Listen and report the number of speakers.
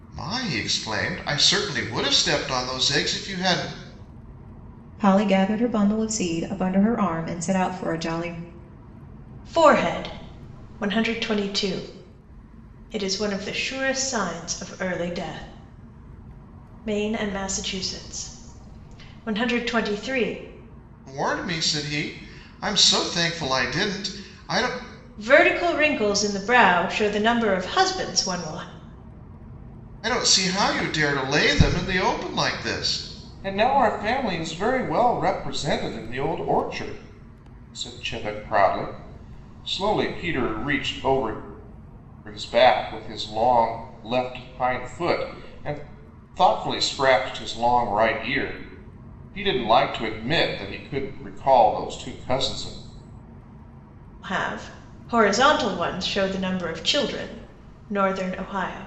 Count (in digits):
3